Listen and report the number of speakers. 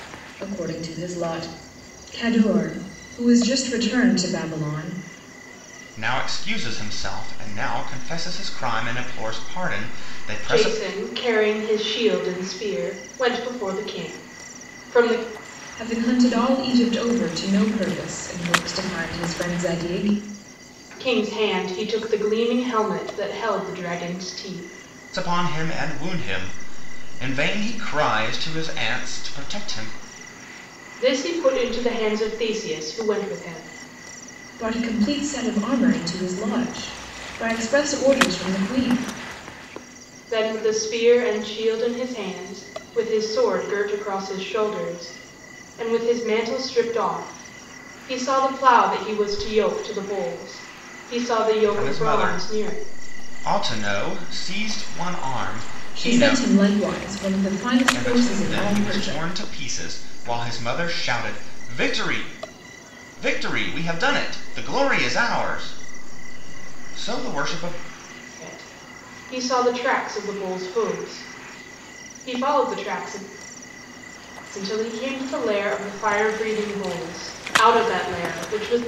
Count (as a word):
three